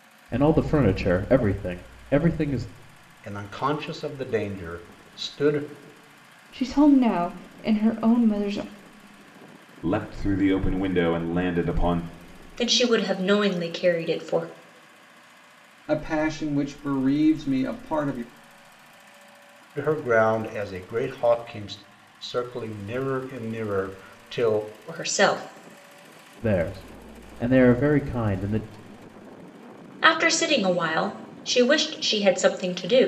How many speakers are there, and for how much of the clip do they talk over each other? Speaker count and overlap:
six, no overlap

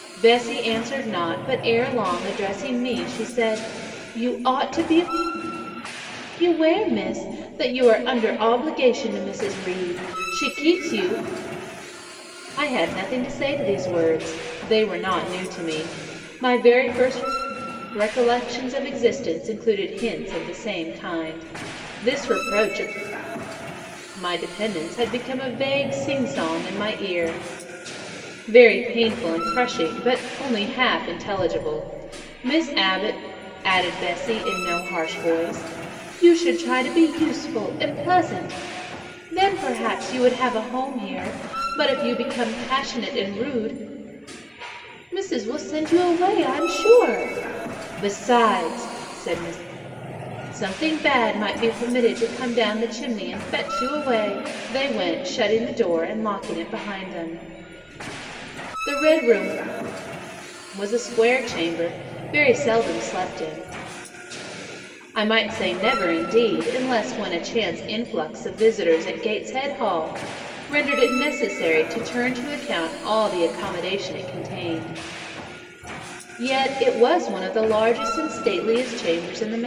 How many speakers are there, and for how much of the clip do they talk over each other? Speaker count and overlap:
one, no overlap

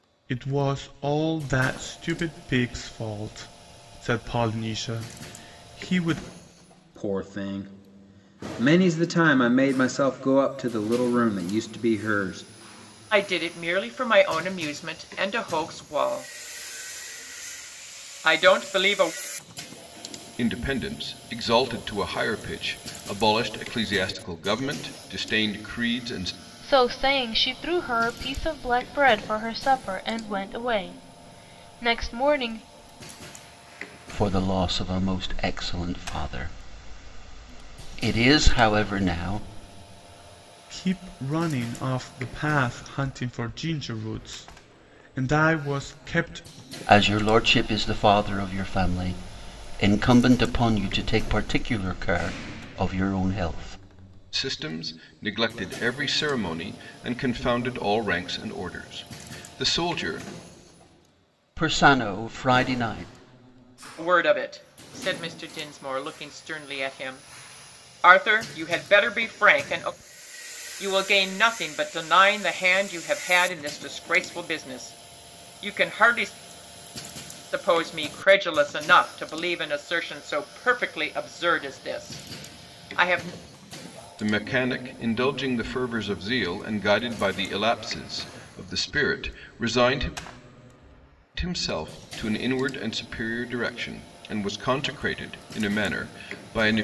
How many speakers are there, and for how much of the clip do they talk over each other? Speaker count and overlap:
six, no overlap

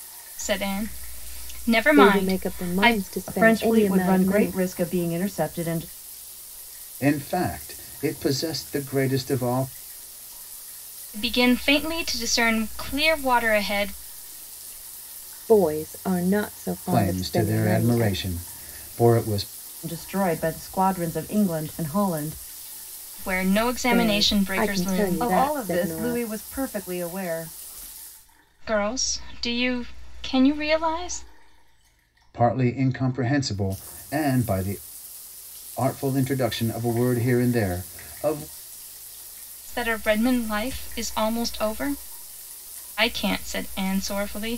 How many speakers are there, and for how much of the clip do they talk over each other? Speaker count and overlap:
four, about 14%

